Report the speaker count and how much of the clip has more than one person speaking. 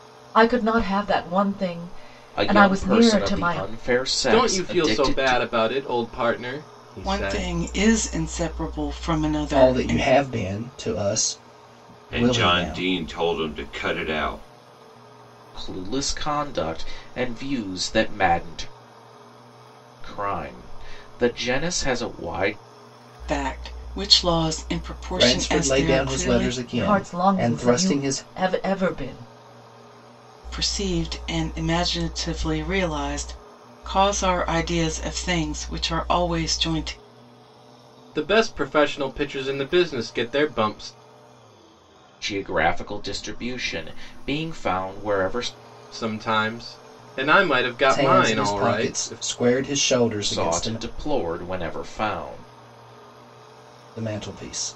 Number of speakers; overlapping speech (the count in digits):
6, about 17%